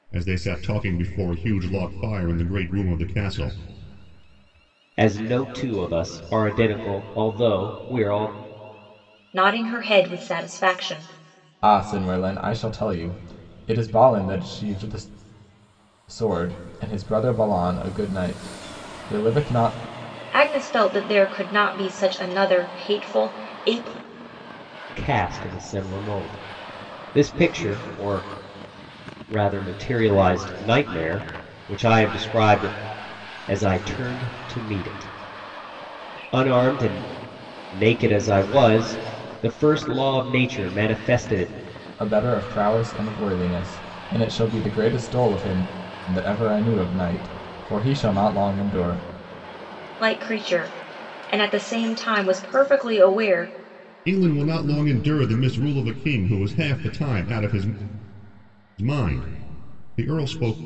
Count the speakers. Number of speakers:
four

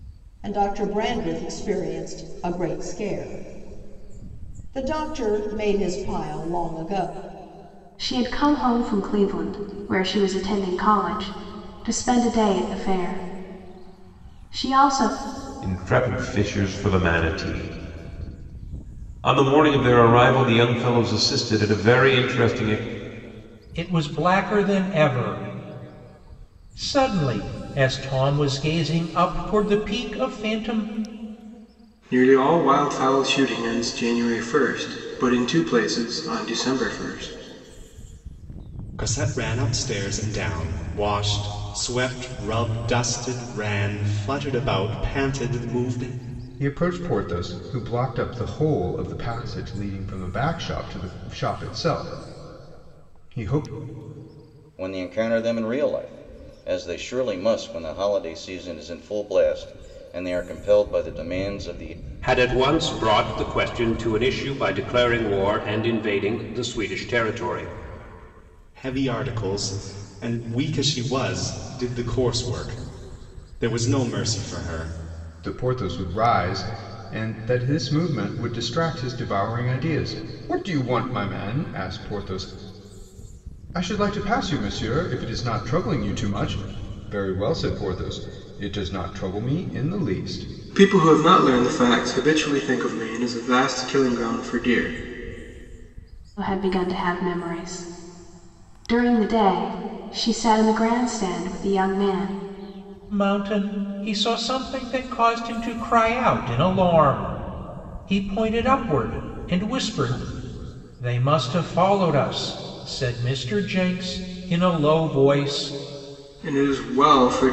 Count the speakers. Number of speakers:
nine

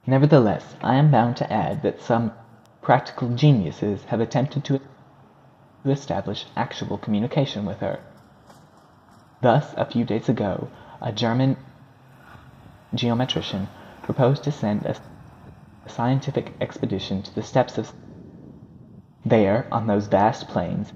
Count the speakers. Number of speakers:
one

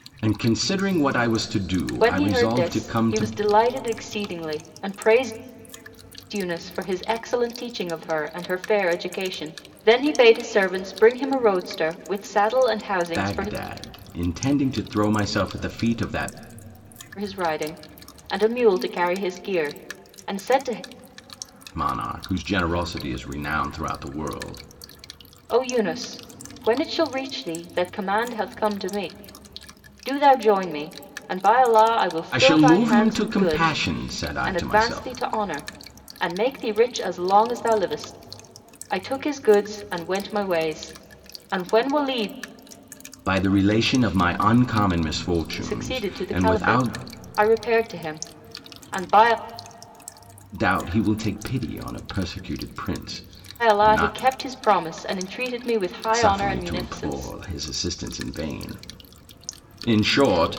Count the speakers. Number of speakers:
two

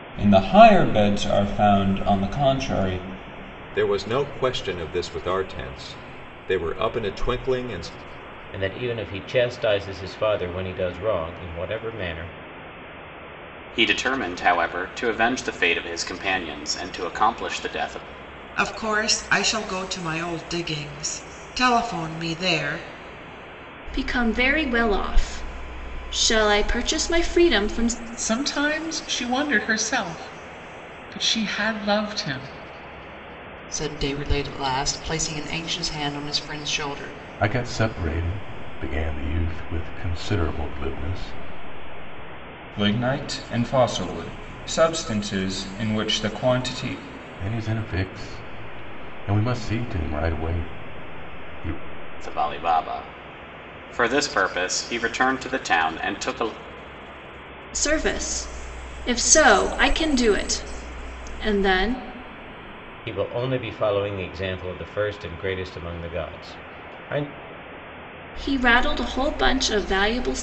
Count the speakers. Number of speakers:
nine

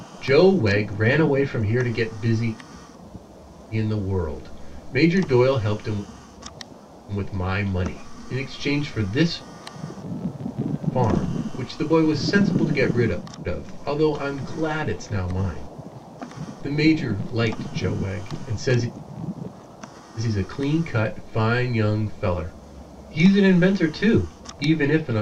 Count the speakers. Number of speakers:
one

